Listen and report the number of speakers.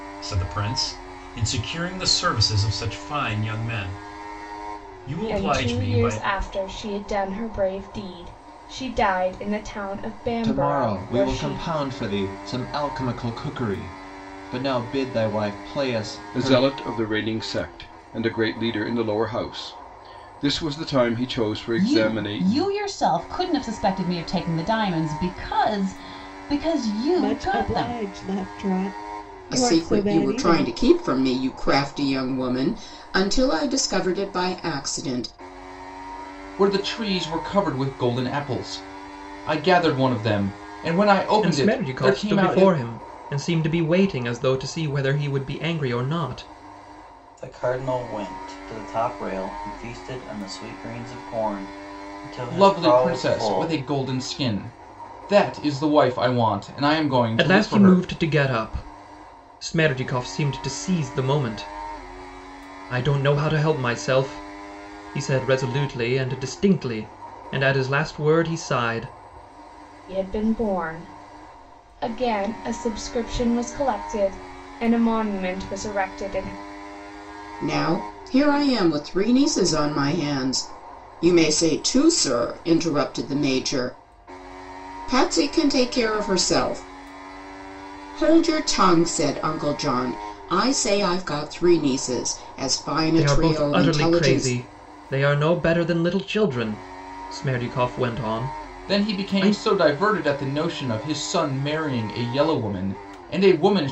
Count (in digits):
10